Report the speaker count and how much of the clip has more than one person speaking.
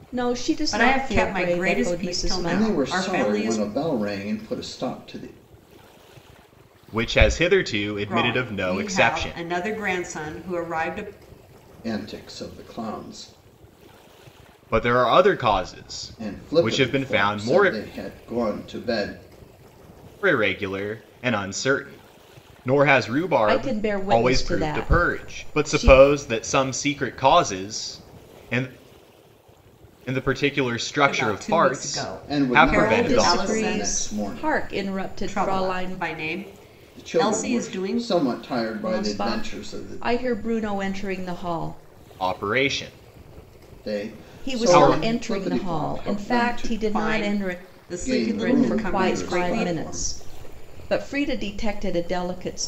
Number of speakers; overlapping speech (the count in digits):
4, about 40%